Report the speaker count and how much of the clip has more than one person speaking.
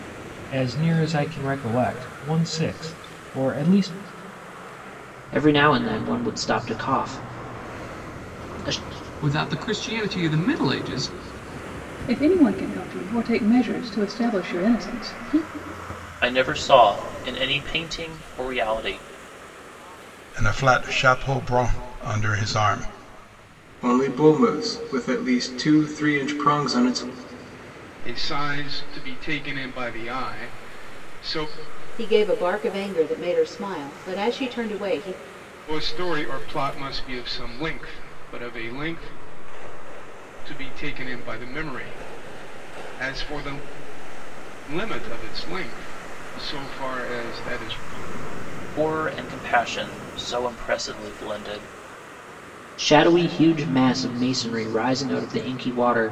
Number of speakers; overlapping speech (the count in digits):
9, no overlap